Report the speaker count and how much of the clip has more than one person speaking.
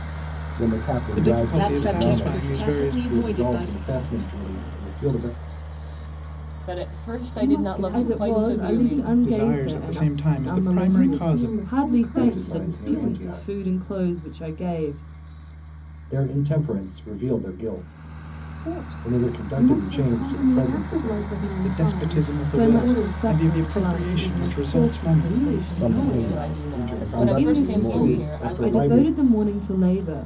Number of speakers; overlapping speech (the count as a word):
seven, about 61%